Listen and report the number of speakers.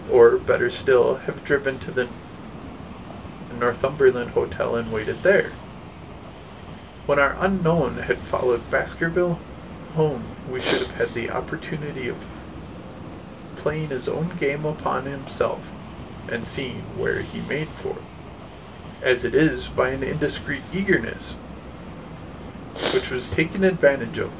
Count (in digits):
1